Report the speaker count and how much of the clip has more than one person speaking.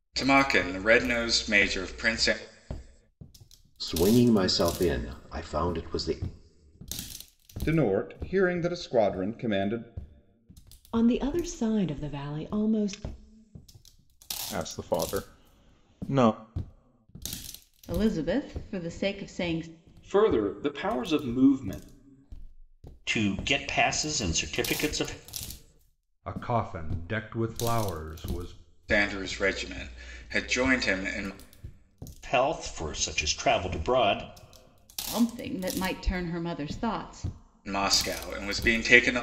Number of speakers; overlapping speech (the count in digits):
9, no overlap